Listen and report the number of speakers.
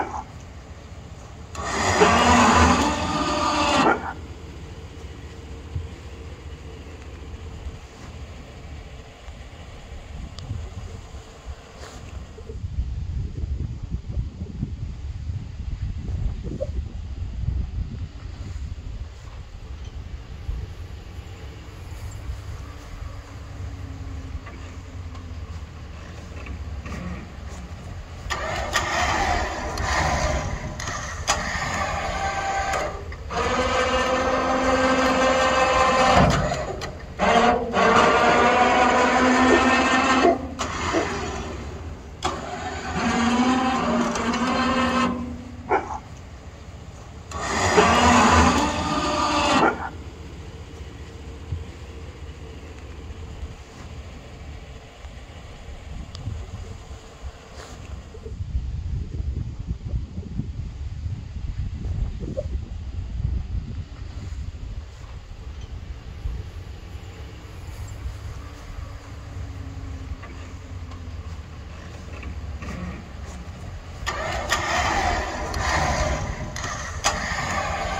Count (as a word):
zero